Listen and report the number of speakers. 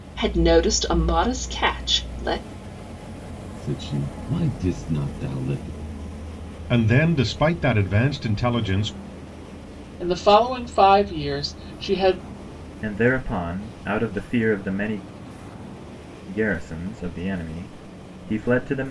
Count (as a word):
five